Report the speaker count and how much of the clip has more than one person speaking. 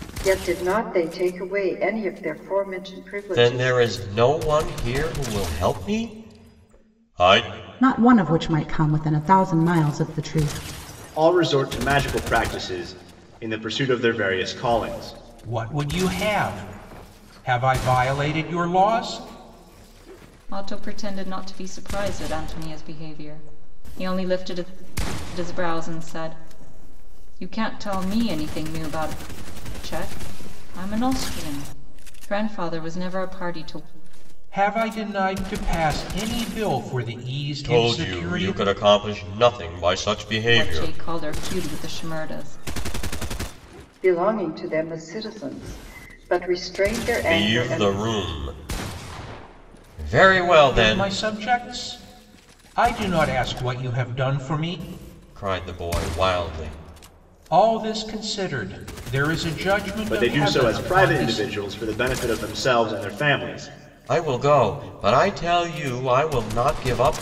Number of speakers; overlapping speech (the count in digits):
6, about 7%